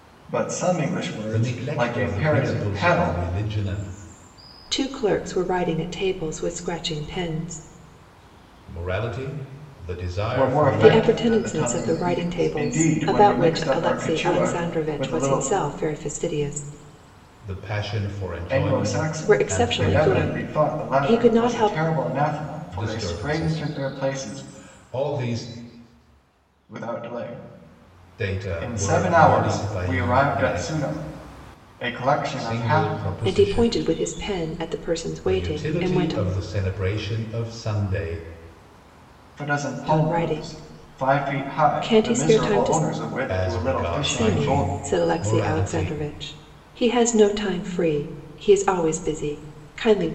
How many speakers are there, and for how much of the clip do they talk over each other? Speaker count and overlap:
three, about 45%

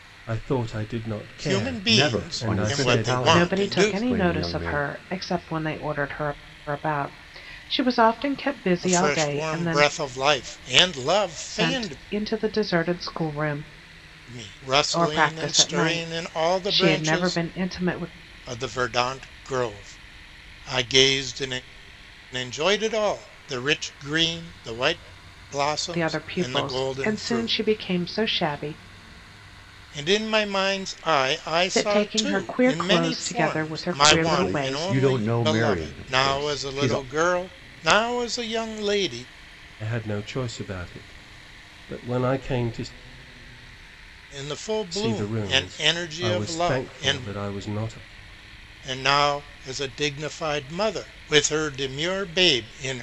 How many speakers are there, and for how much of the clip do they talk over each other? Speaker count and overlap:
four, about 32%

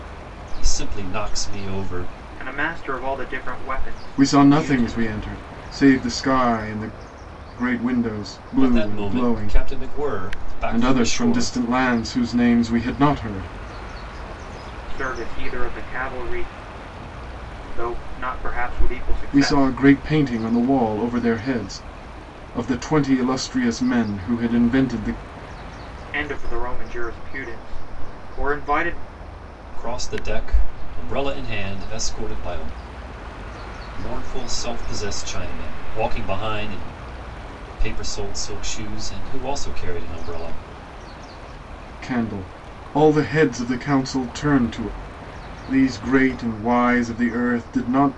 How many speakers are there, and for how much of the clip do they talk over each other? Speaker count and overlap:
three, about 7%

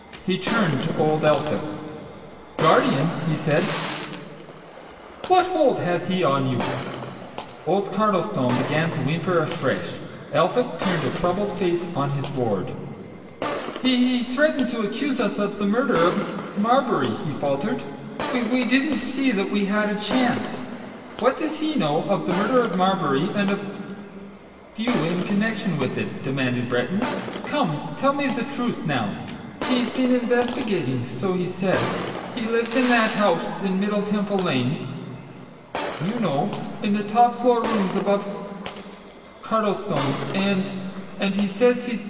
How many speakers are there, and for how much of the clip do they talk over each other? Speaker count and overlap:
one, no overlap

